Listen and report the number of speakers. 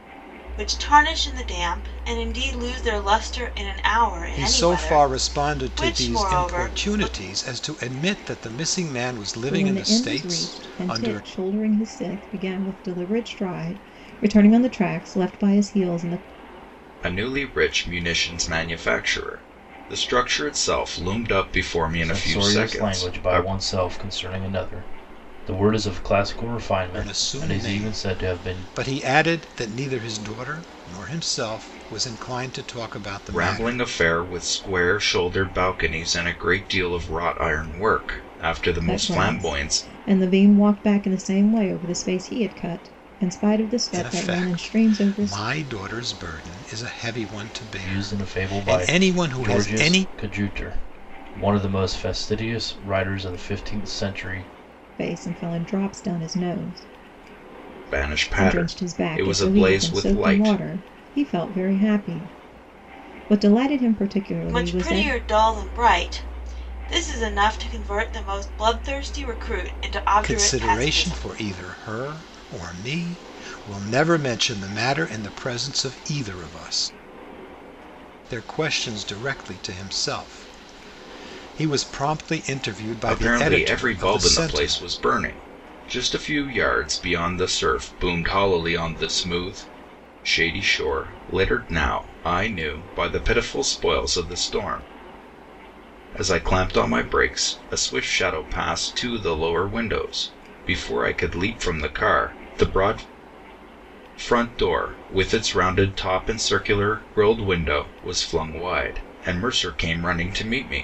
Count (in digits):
5